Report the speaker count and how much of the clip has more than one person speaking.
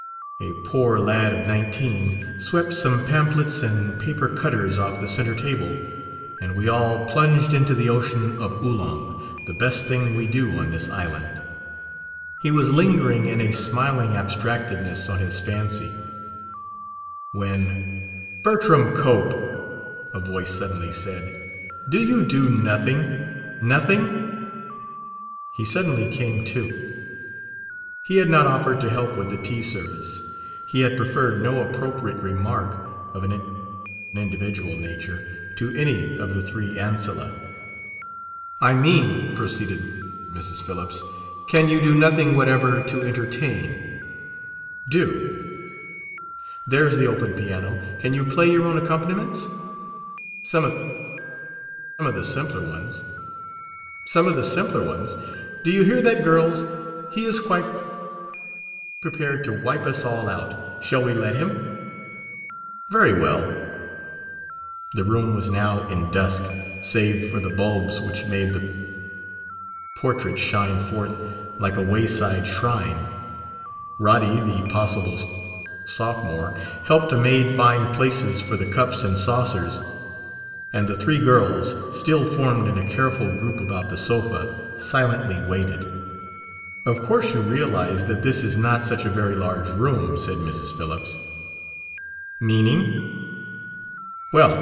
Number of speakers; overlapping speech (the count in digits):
1, no overlap